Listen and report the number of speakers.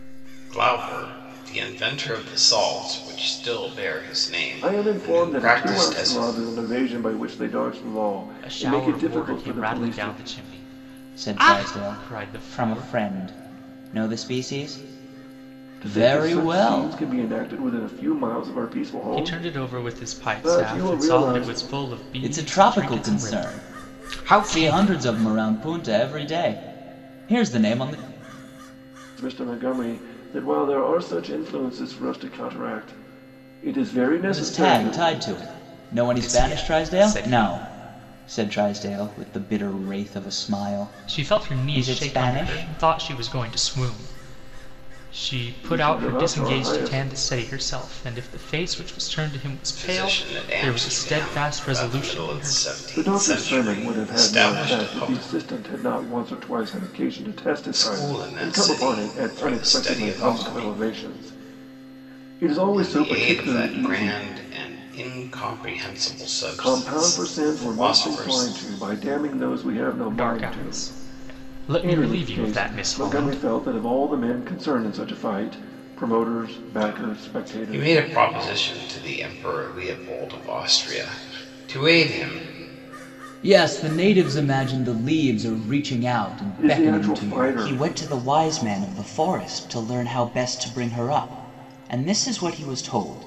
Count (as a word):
four